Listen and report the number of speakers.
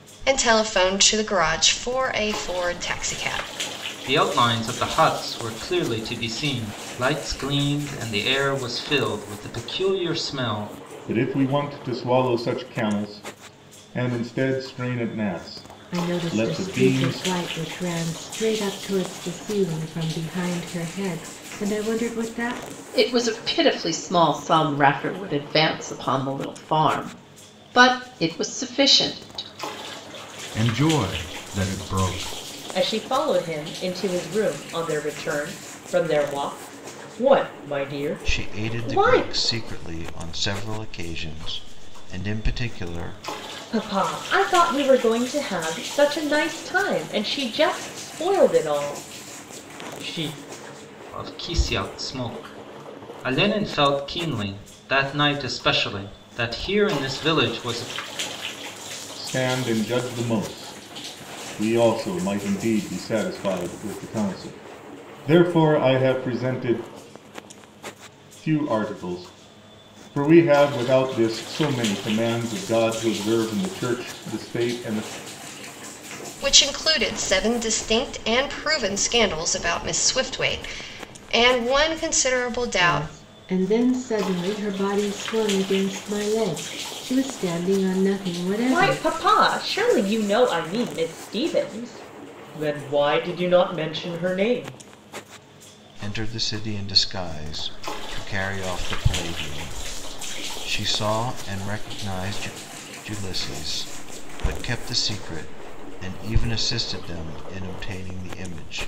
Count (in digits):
8